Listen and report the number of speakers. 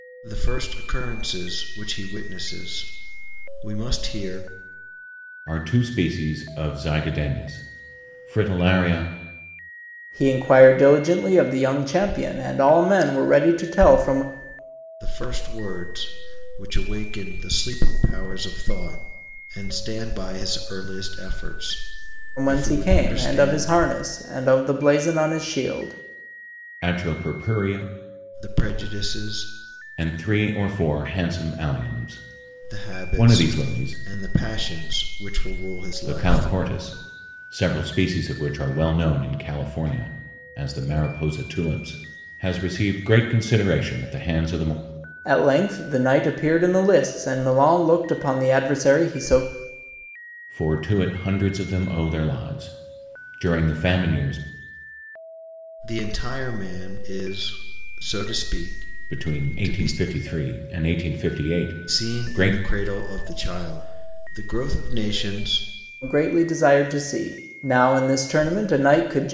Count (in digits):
3